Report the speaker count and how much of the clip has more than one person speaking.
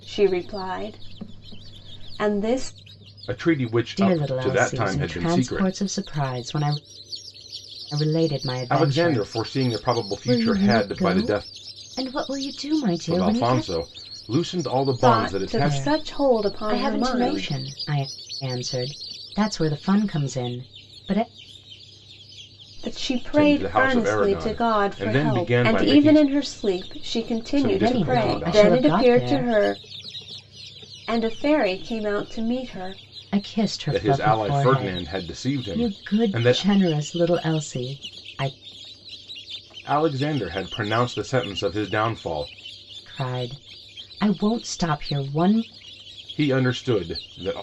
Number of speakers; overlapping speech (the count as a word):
three, about 33%